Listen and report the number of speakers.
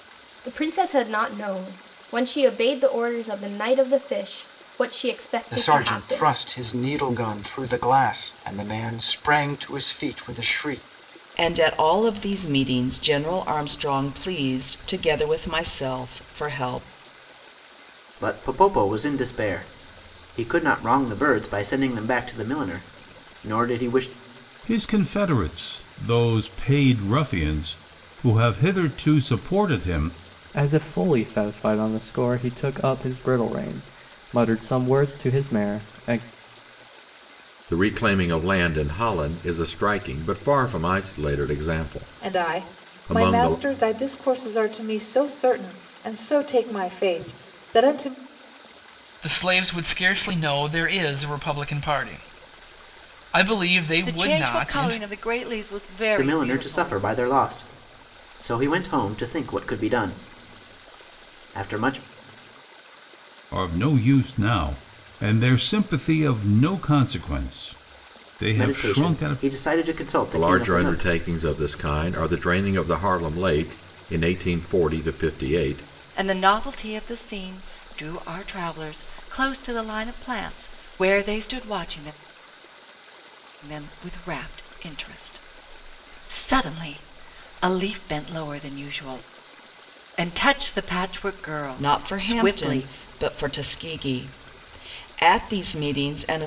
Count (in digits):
10